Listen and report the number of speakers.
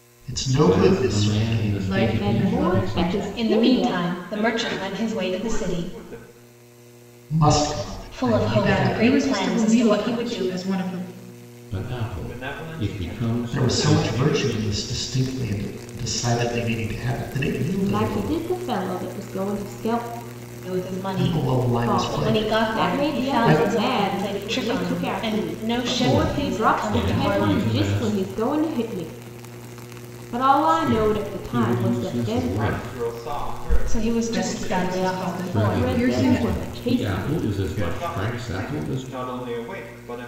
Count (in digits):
6